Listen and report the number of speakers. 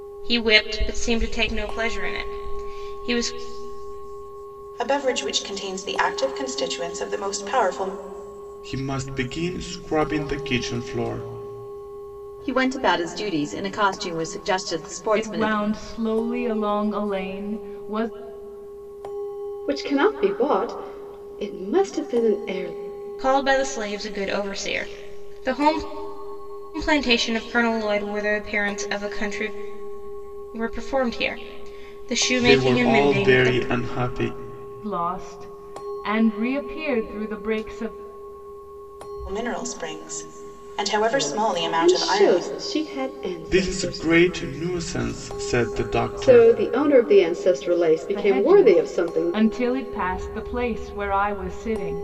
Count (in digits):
6